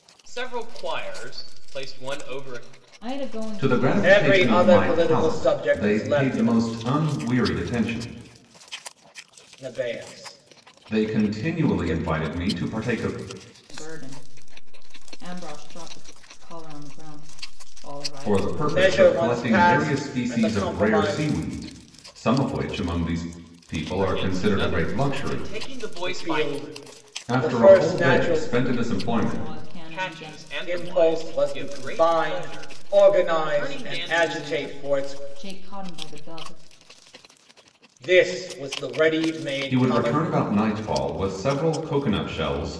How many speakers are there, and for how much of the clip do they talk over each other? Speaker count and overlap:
4, about 40%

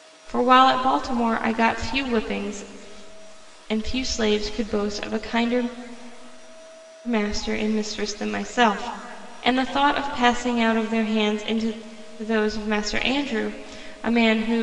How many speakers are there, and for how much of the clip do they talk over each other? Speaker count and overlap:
1, no overlap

